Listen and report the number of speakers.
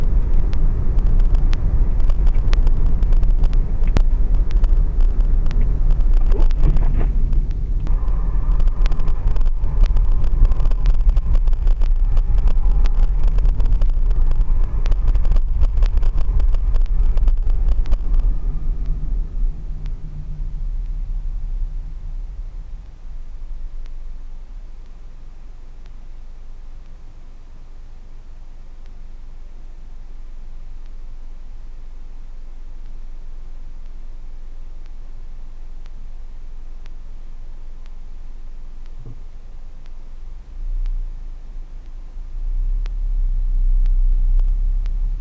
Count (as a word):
zero